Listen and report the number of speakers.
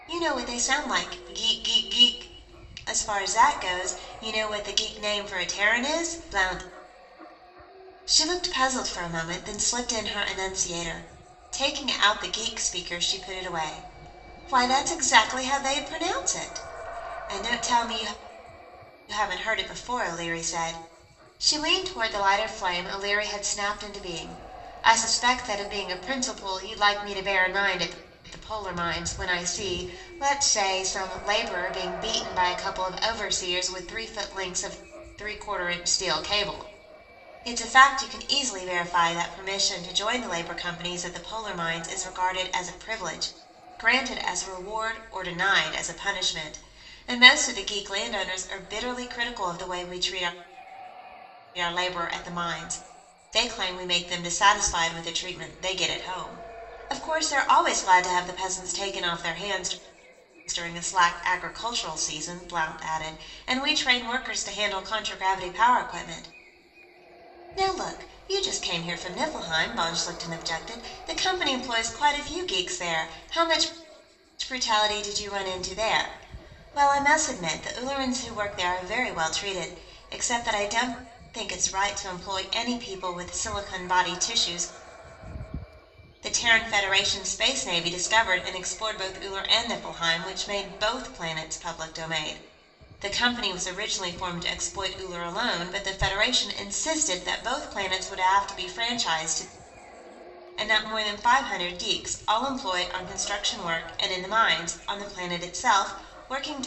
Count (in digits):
1